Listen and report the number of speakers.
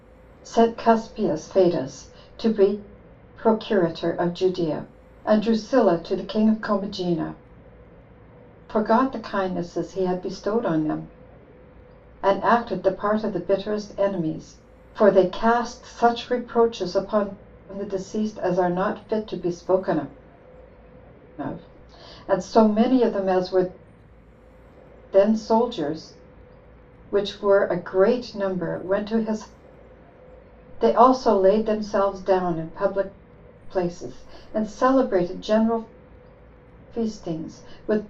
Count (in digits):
1